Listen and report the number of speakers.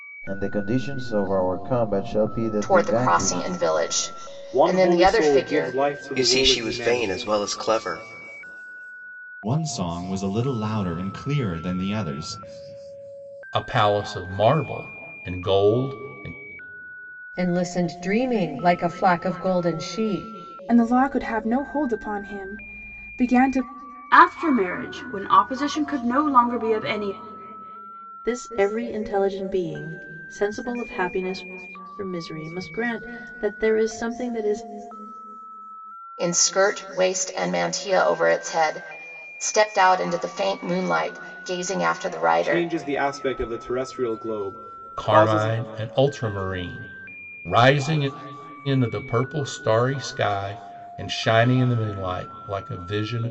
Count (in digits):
10